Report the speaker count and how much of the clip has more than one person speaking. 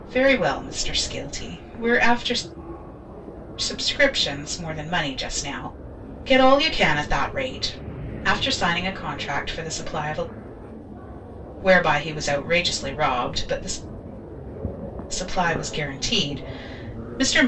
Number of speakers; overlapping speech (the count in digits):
1, no overlap